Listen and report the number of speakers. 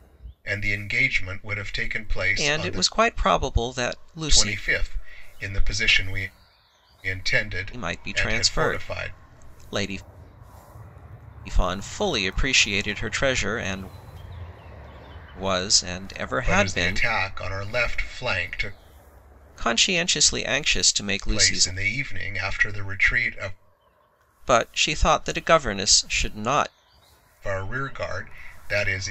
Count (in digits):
2